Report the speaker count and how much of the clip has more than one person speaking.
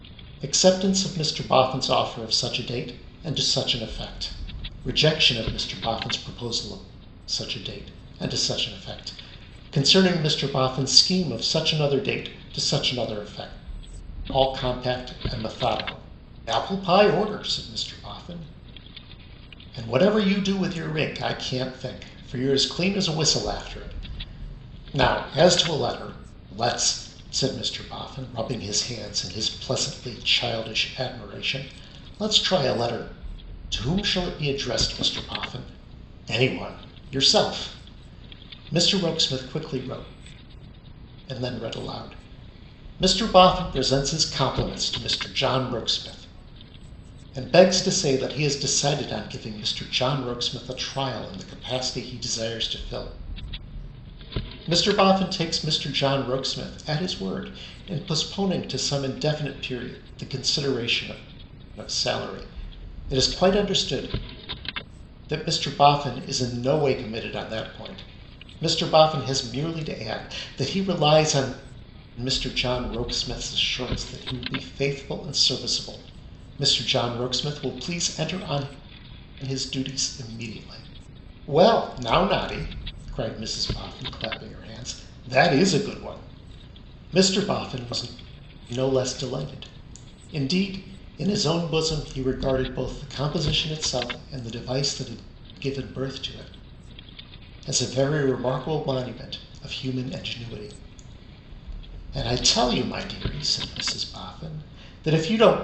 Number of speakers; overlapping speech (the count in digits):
1, no overlap